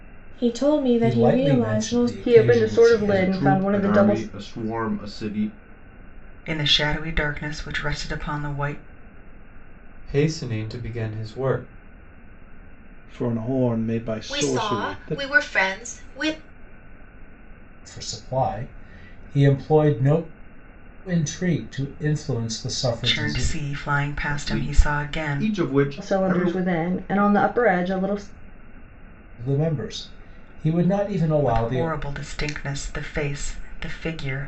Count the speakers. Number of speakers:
8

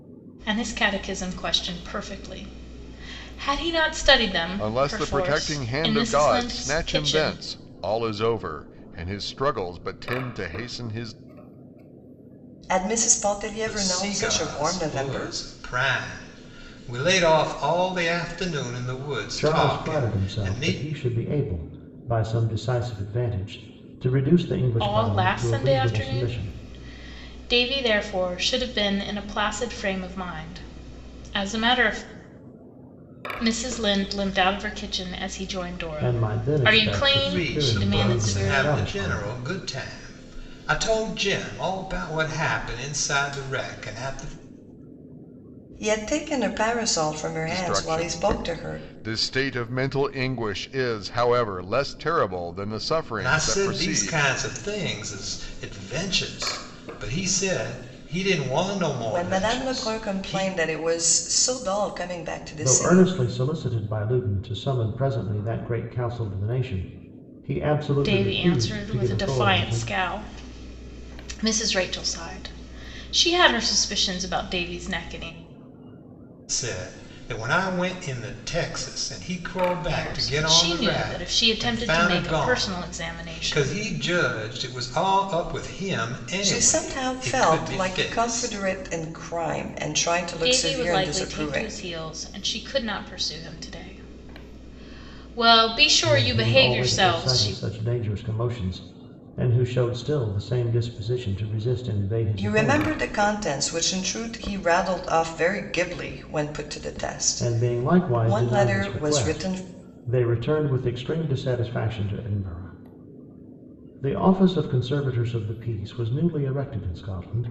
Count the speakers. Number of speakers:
5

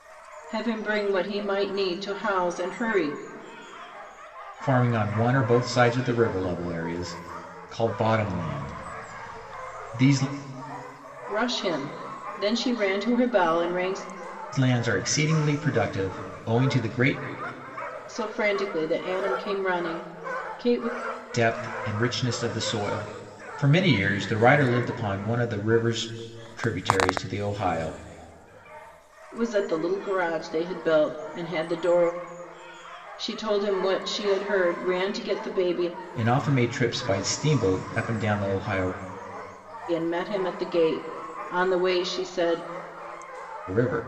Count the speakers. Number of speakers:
2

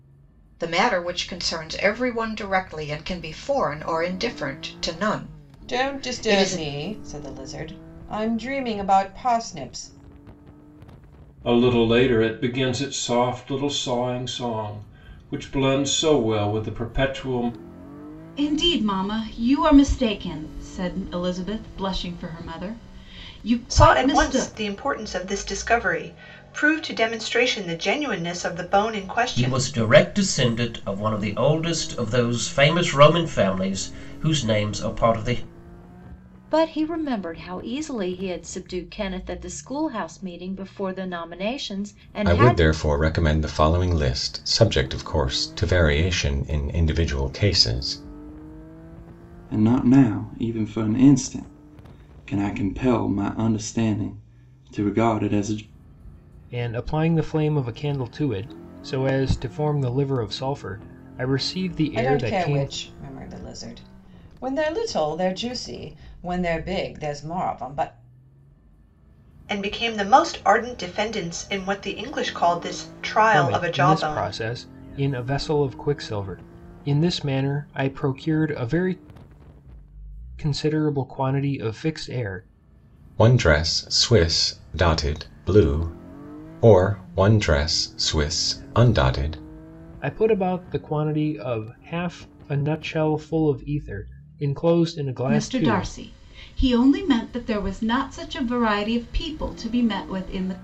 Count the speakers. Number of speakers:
10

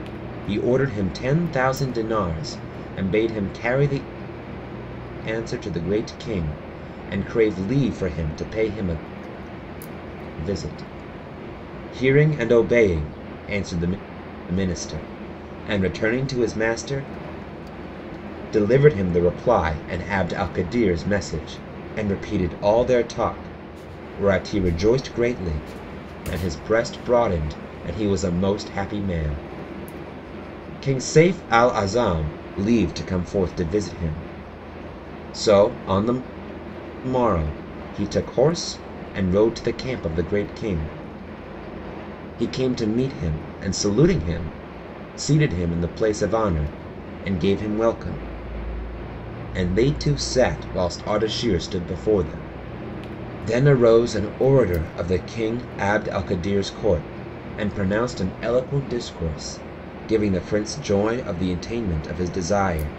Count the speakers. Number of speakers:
1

